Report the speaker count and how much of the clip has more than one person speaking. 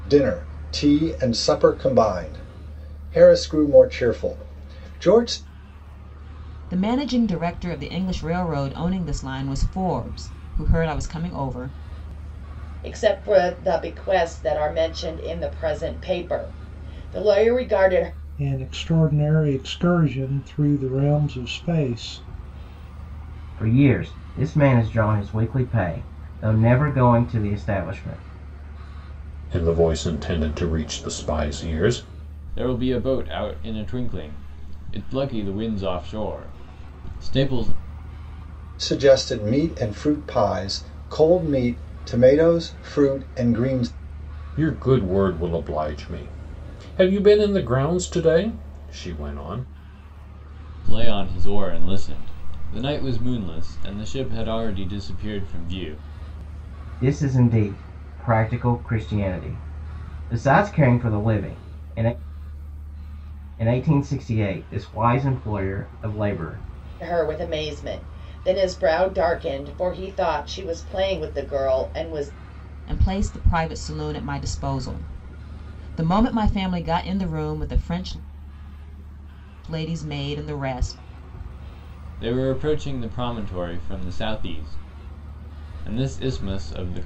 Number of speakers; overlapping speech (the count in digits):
7, no overlap